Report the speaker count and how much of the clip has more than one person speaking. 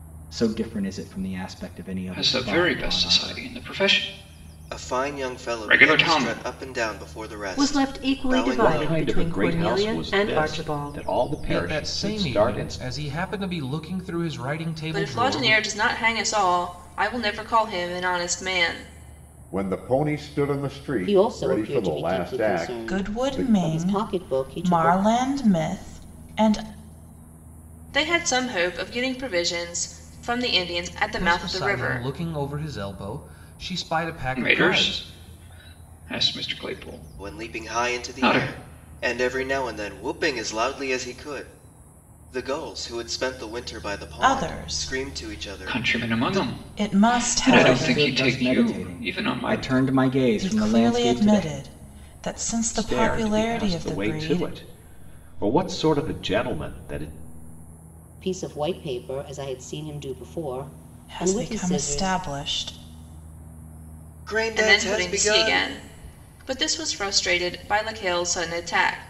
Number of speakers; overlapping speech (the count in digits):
10, about 38%